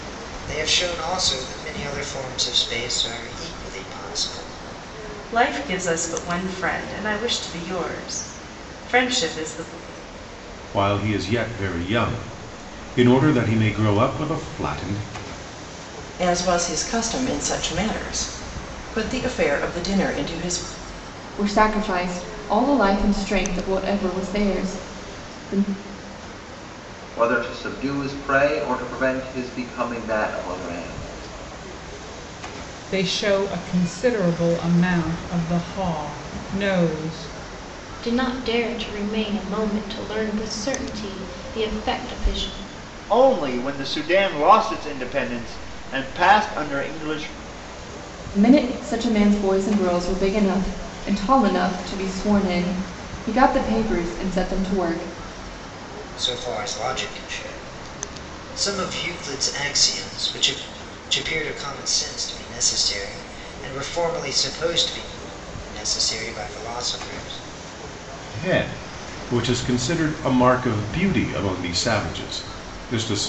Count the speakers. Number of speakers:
9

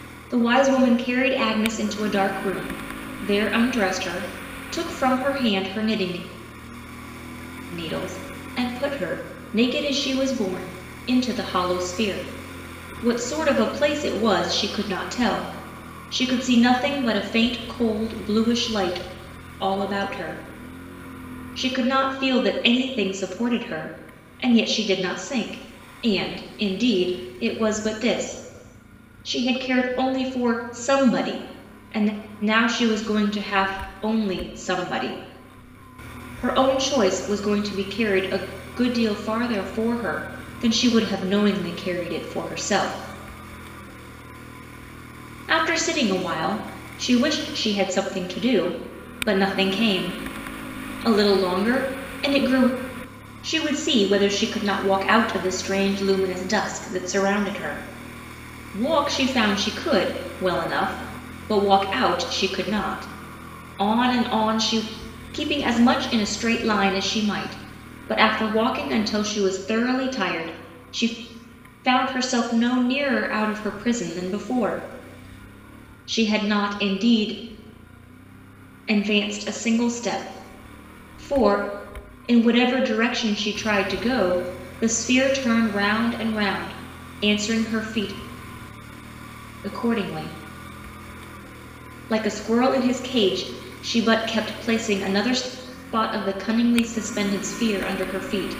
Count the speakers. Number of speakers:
1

